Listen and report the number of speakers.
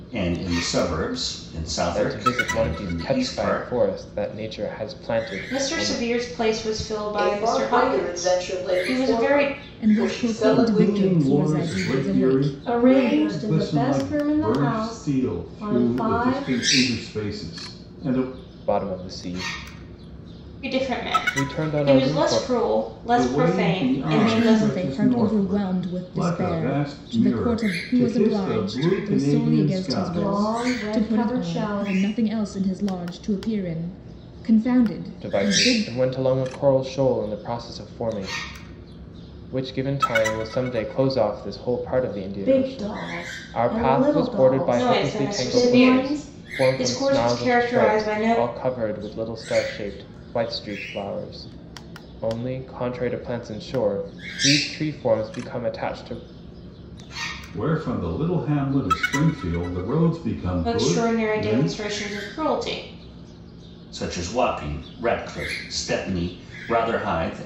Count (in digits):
7